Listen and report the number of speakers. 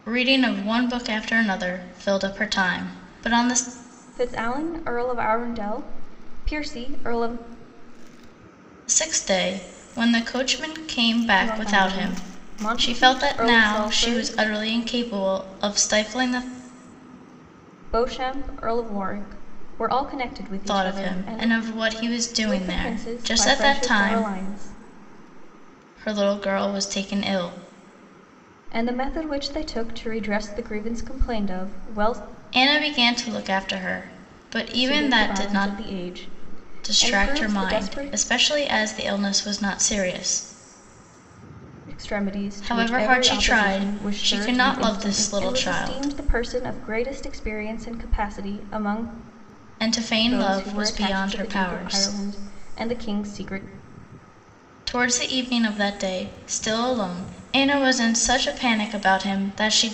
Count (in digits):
2